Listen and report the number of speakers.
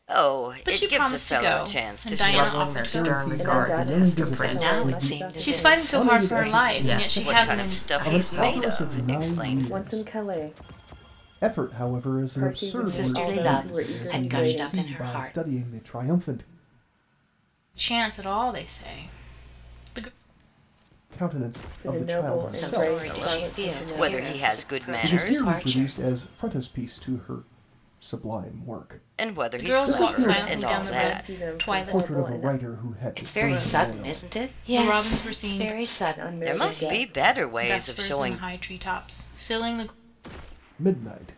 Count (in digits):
6